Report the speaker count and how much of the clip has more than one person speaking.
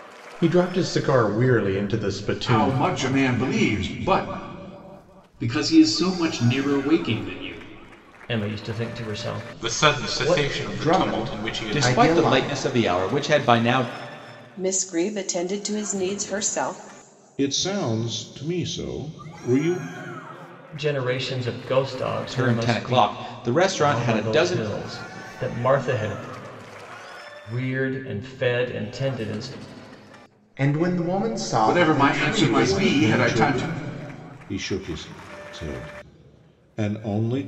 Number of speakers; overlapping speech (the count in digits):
9, about 19%